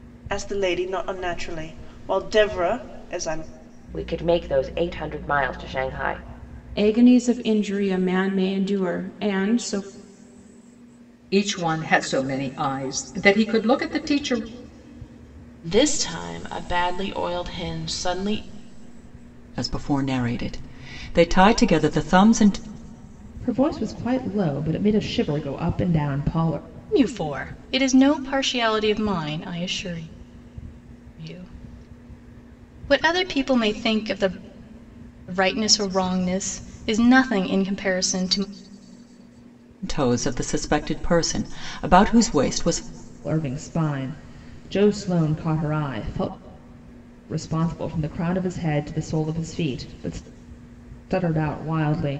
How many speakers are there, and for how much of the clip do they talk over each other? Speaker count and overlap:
8, no overlap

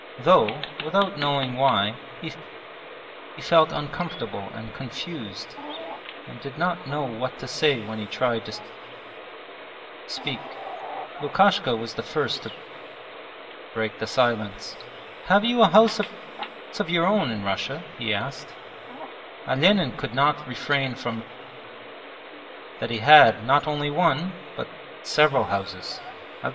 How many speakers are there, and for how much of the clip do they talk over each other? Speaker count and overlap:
1, no overlap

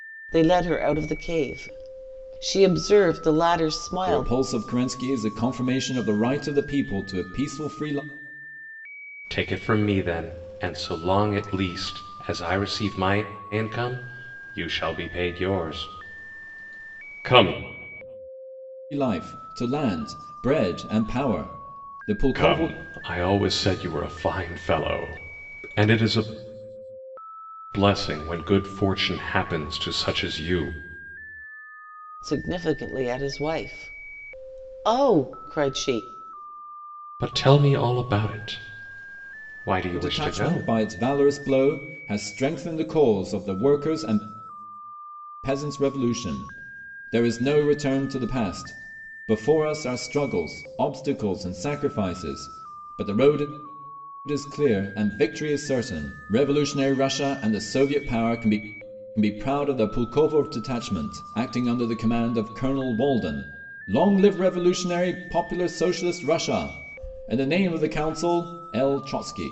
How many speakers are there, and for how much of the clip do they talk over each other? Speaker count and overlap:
3, about 2%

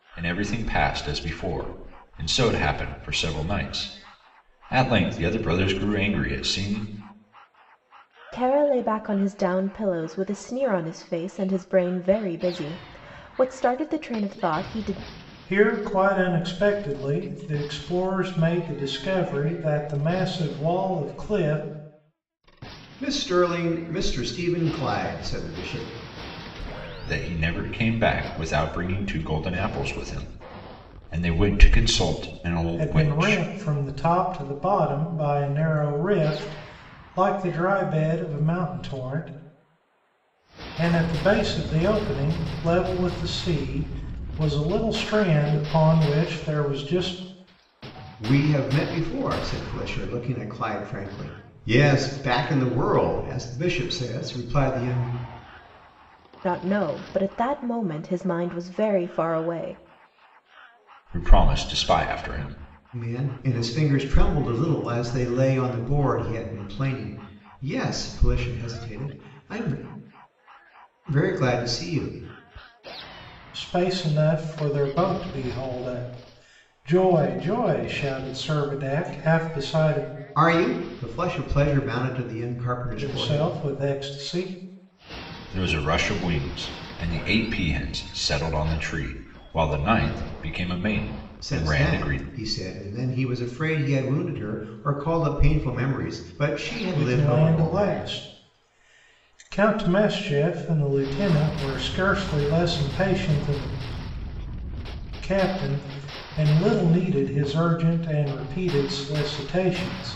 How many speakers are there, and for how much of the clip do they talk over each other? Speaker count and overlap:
4, about 3%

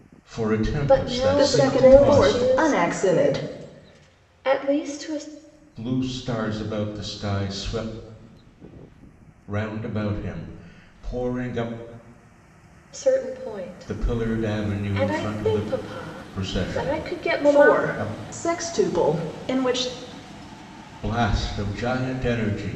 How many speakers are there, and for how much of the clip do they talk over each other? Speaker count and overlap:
3, about 28%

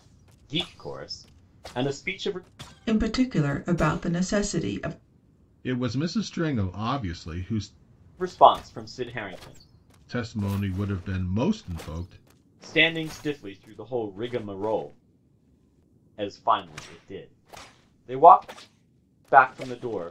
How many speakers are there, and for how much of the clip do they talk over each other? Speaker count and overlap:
3, no overlap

